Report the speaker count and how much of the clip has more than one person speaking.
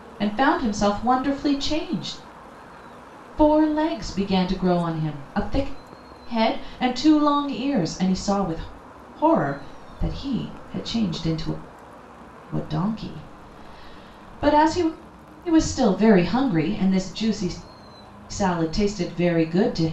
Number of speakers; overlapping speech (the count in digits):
1, no overlap